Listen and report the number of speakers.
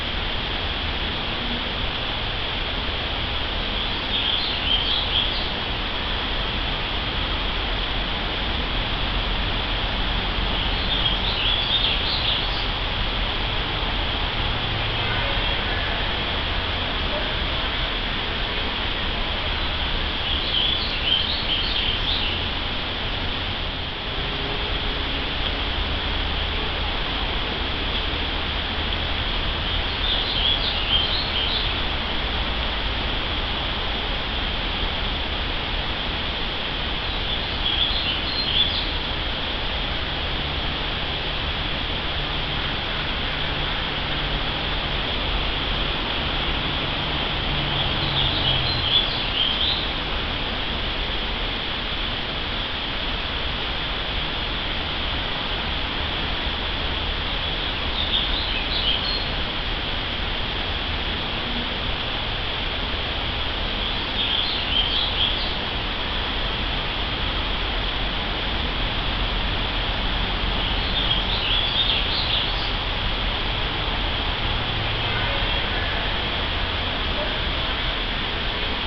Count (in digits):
0